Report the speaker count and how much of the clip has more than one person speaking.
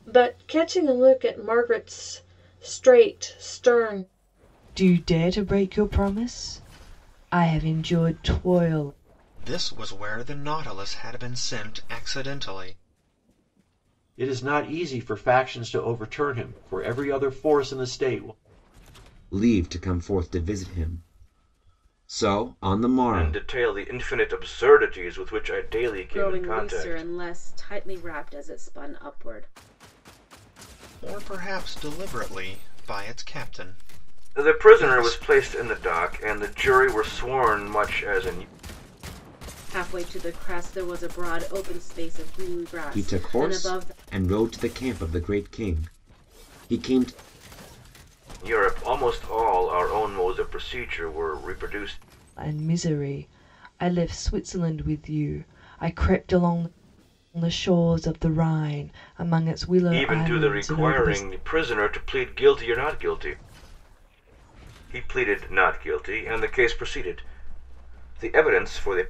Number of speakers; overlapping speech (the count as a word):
seven, about 7%